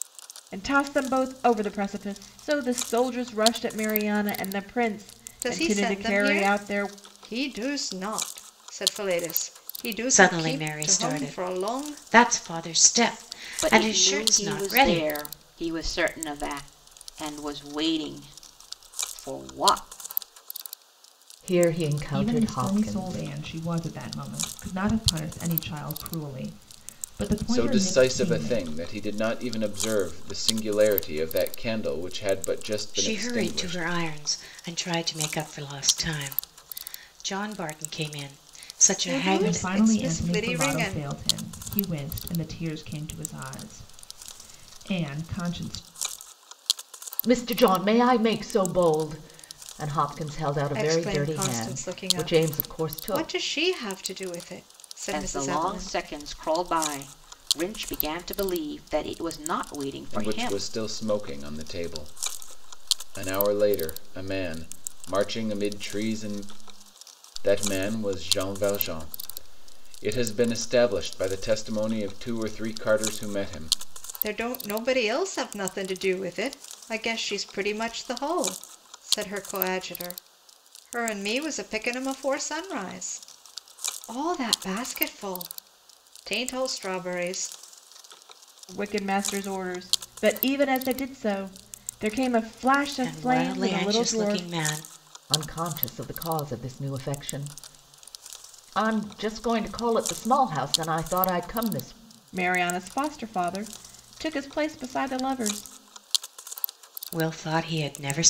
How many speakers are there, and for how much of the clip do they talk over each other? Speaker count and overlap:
7, about 15%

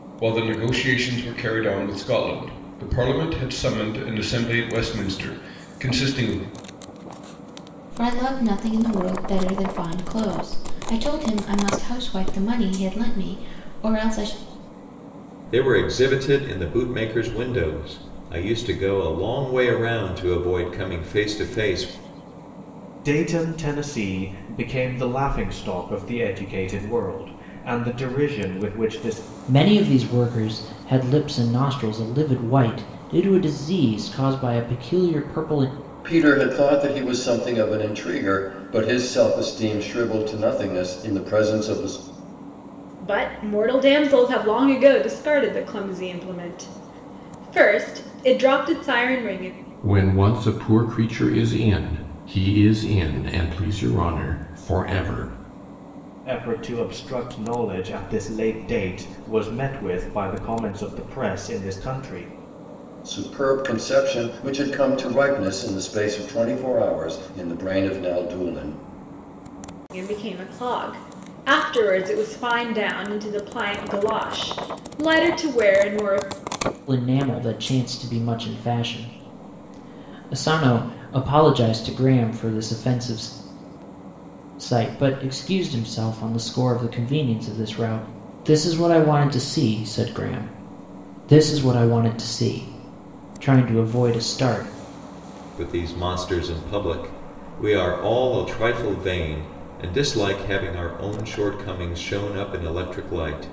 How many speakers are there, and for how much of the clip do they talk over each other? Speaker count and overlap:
8, no overlap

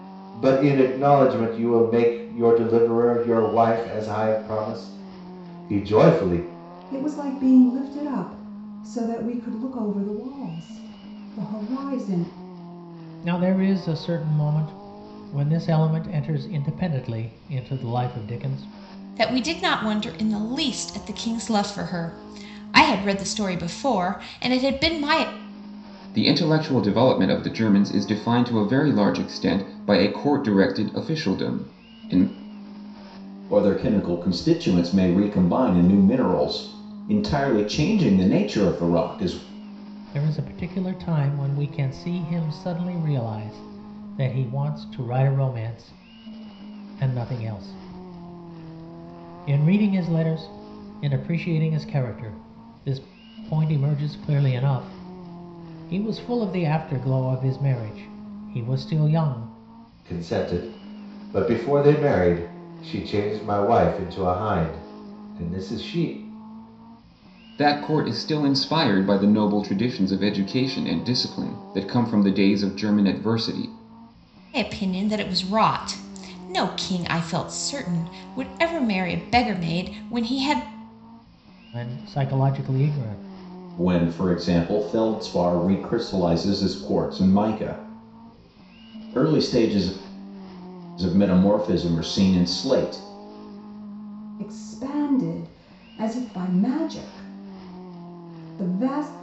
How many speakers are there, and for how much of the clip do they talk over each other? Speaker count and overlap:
6, no overlap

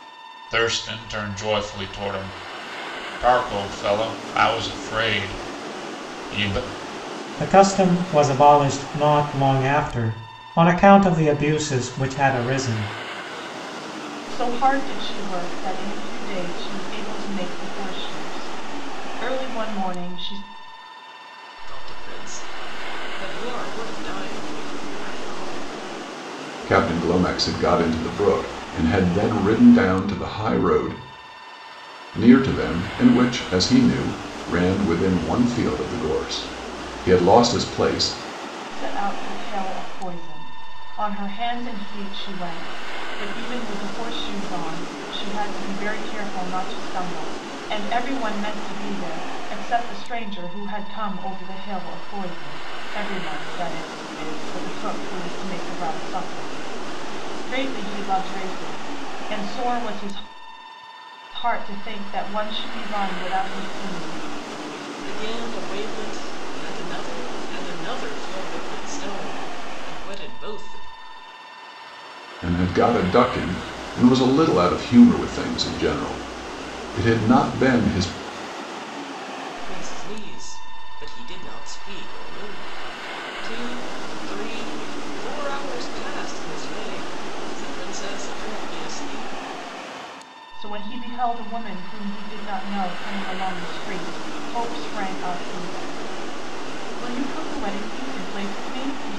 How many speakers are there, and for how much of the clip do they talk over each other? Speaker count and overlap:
5, no overlap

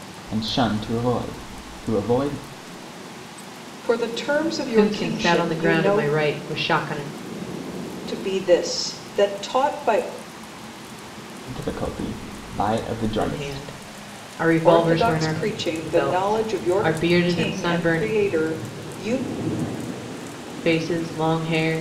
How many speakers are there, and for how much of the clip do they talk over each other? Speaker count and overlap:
3, about 22%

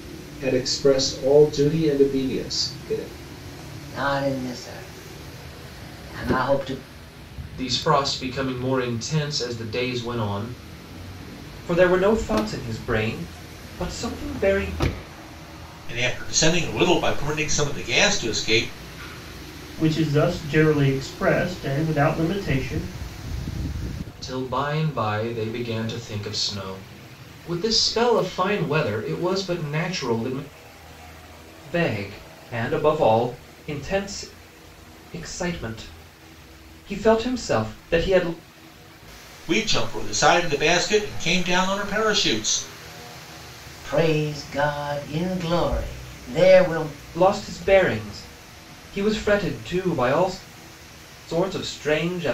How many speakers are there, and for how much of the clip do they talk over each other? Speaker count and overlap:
6, no overlap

